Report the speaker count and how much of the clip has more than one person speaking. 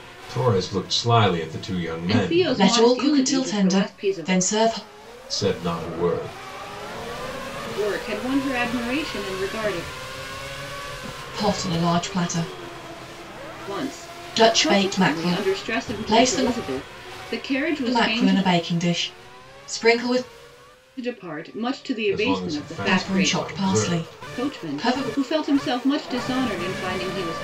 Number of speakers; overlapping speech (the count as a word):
three, about 30%